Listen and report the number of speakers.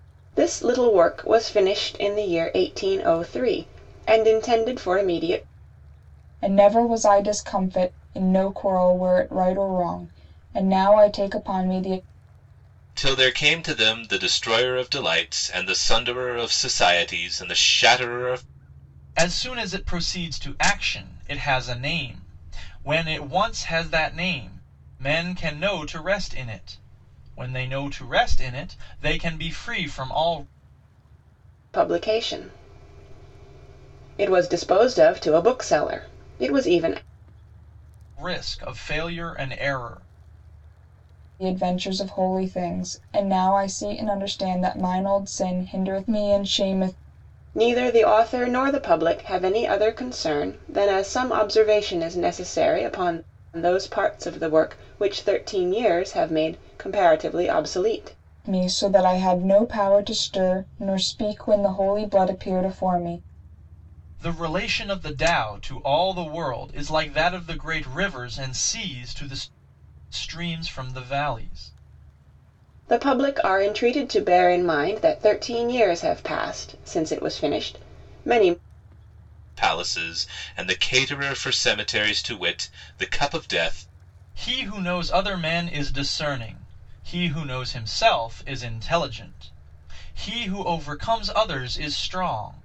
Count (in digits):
4